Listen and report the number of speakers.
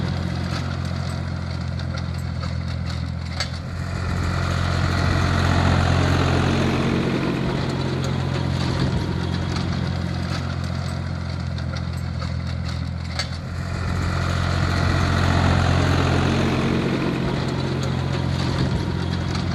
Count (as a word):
zero